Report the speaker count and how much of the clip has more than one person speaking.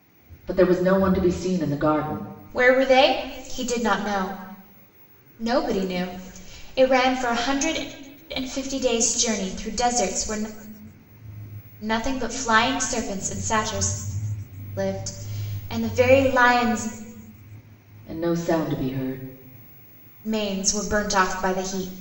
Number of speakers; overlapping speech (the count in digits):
2, no overlap